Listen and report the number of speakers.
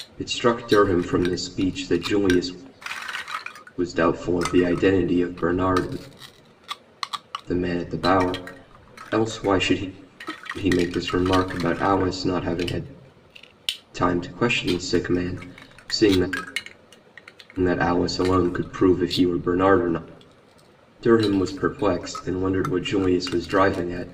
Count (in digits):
1